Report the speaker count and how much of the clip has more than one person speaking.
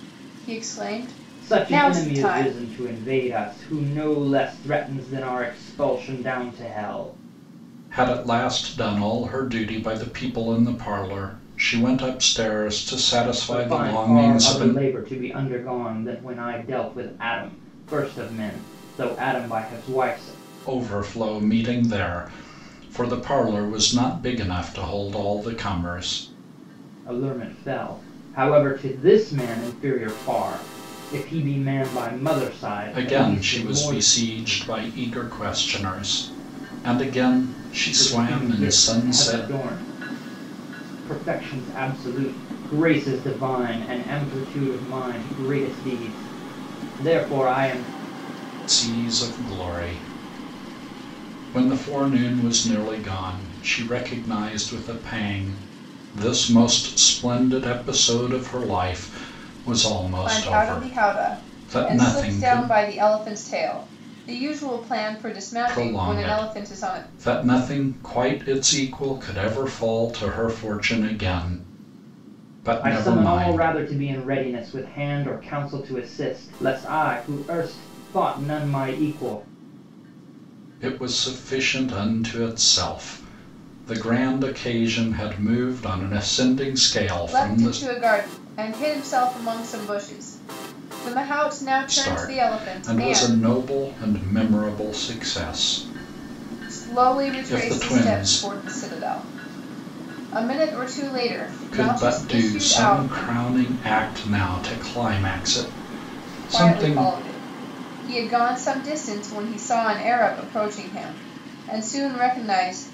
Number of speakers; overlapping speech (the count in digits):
3, about 15%